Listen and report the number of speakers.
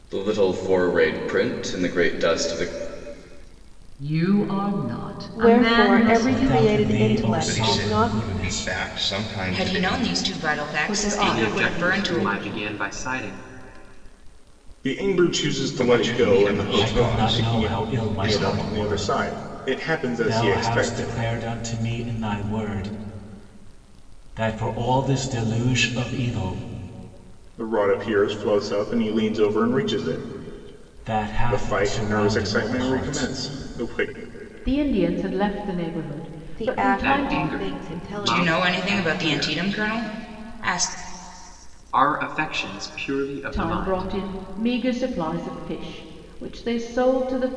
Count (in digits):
9